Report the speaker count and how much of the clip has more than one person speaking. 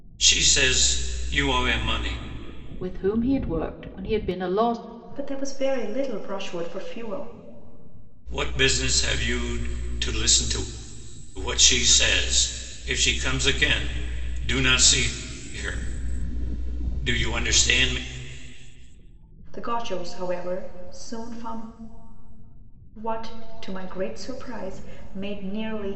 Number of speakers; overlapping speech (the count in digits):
3, no overlap